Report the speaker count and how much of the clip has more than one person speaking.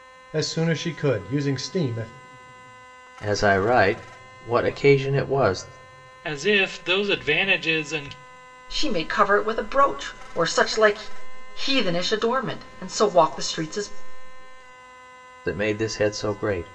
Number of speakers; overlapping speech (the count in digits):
4, no overlap